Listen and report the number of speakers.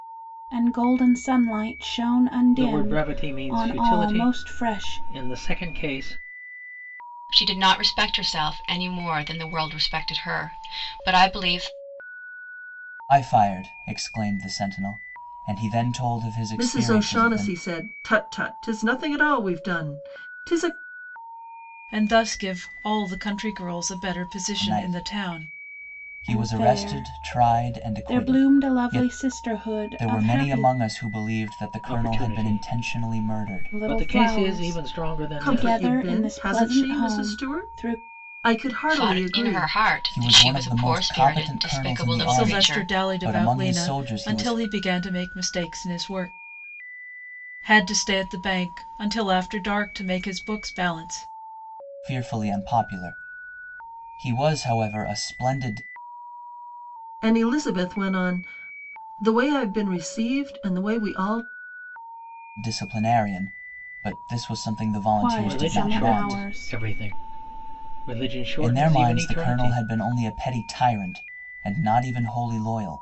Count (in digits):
6